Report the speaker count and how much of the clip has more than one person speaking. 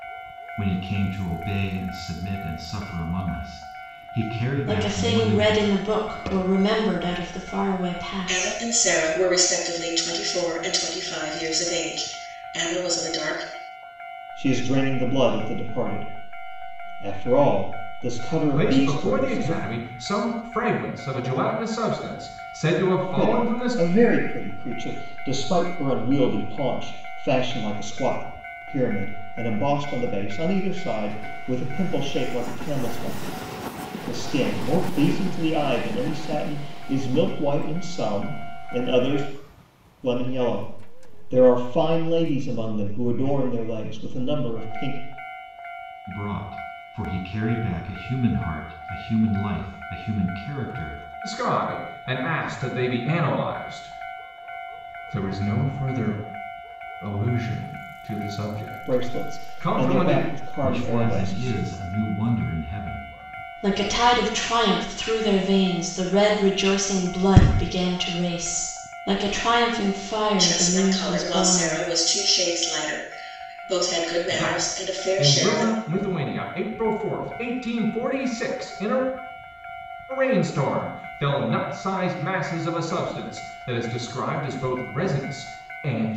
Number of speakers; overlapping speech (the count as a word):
five, about 10%